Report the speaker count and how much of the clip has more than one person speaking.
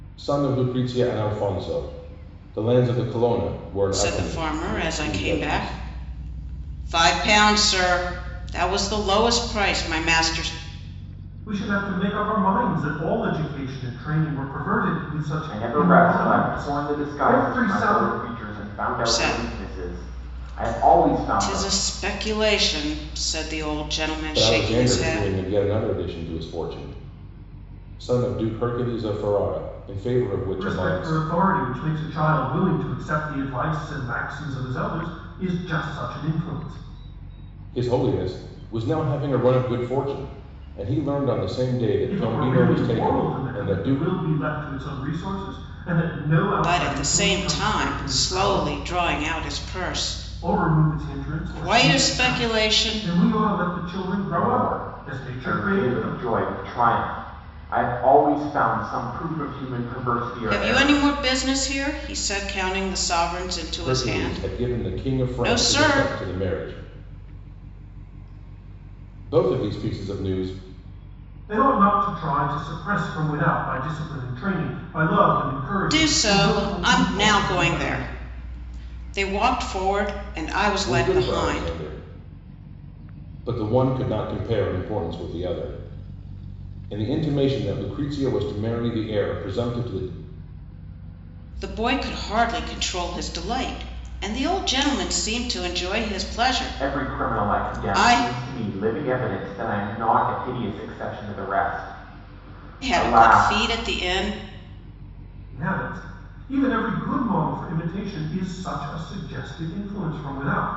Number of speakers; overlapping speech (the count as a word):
four, about 24%